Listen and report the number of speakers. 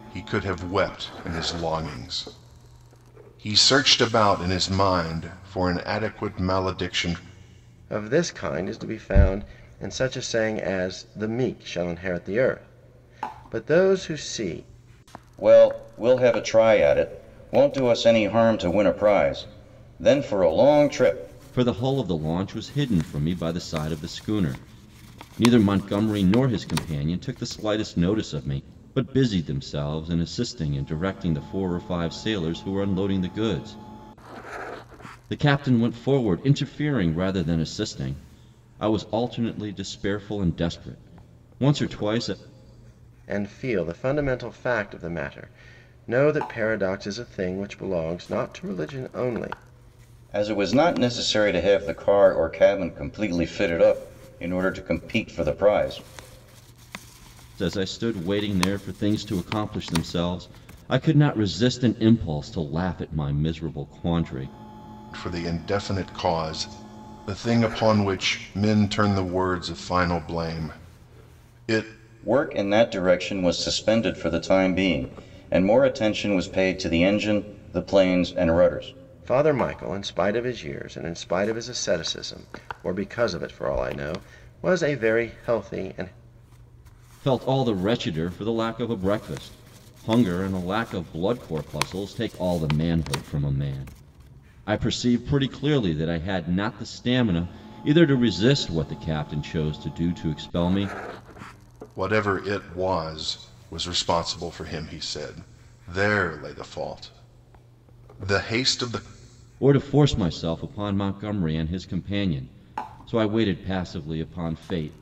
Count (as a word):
four